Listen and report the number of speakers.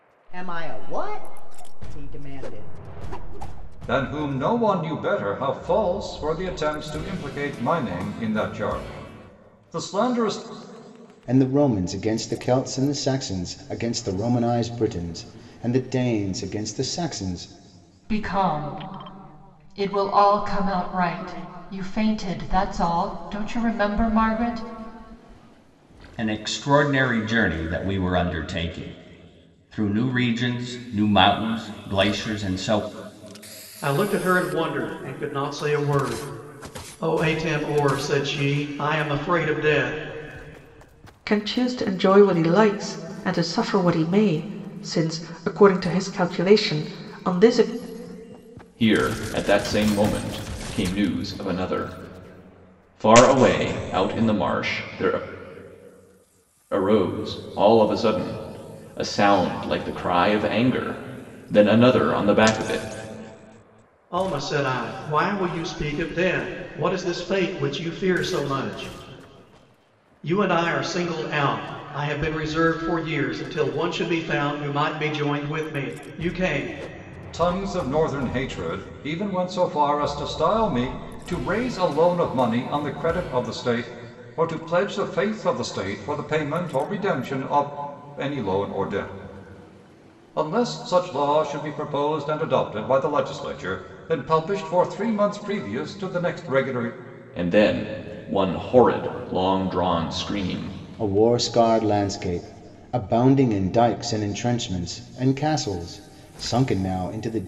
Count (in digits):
8